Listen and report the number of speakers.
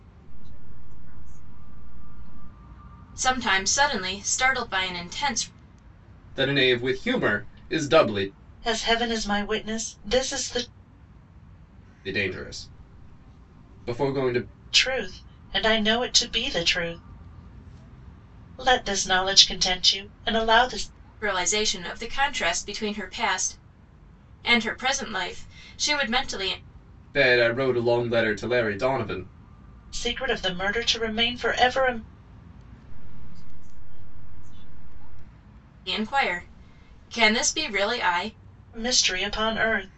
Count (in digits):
4